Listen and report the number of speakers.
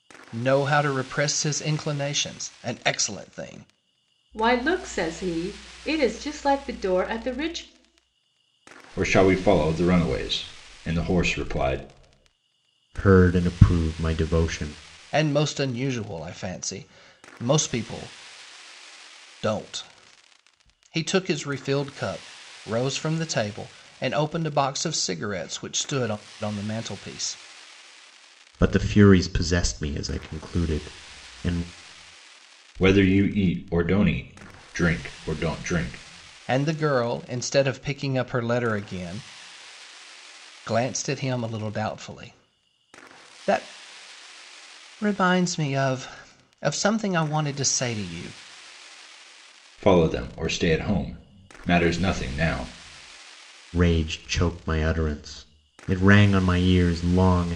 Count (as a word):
four